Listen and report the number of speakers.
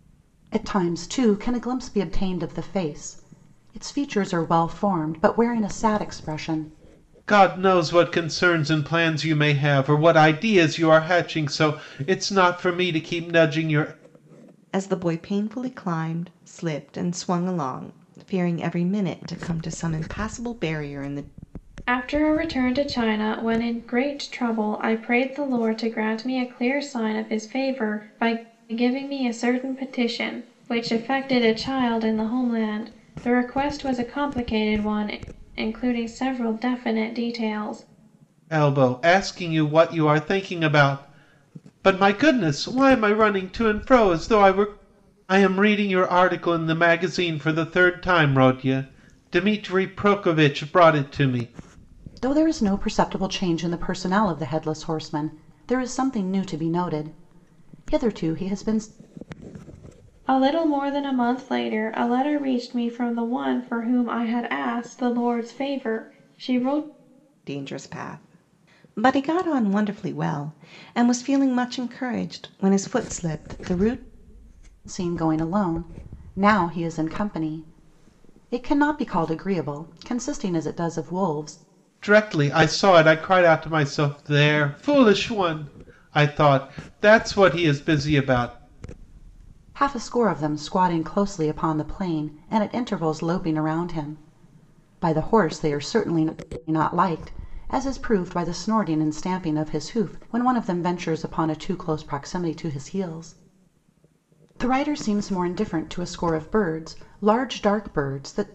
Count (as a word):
four